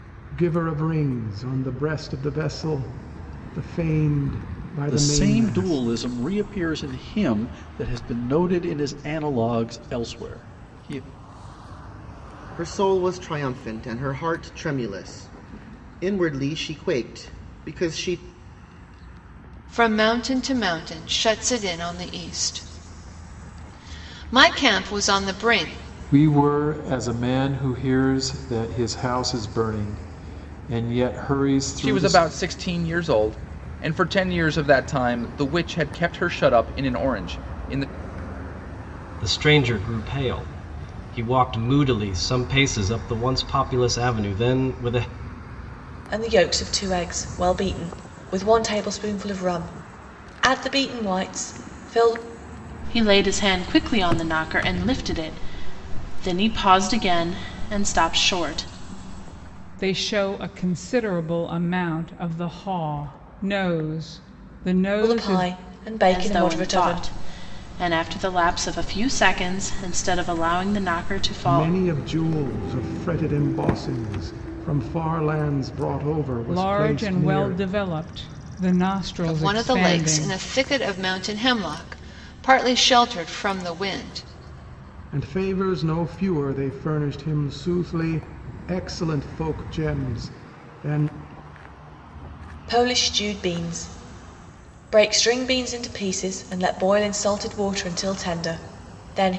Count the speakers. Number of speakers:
10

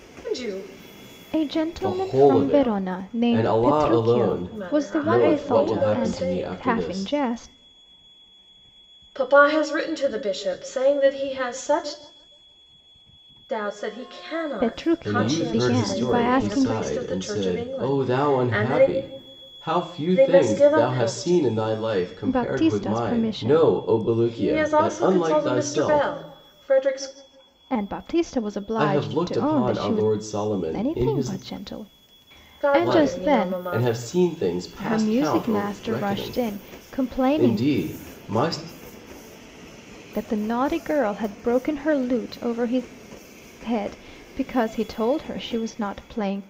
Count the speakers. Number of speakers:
3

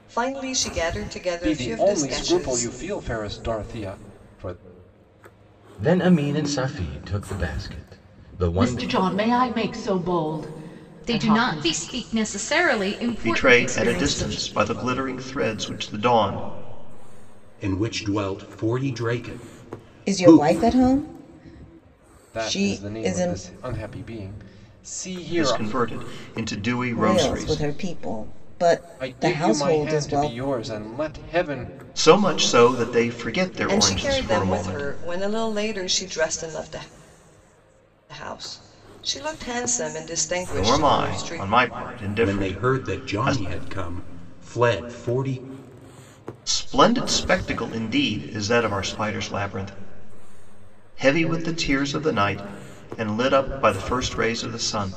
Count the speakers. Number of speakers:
8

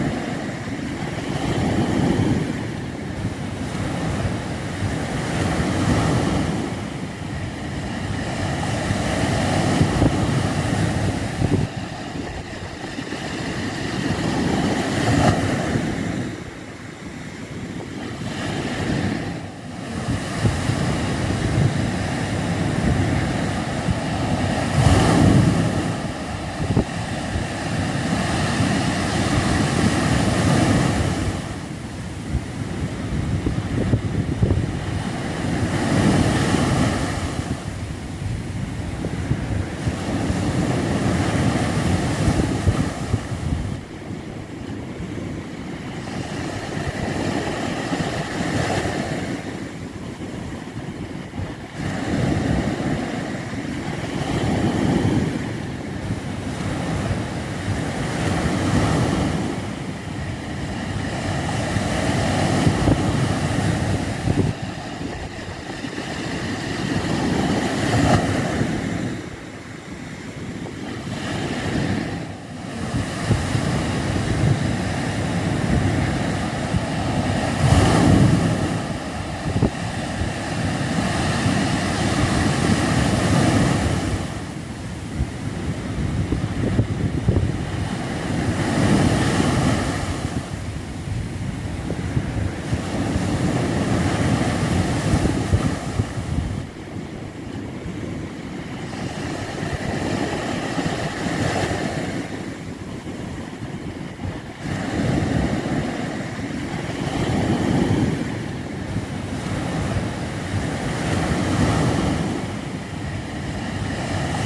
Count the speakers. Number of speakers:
0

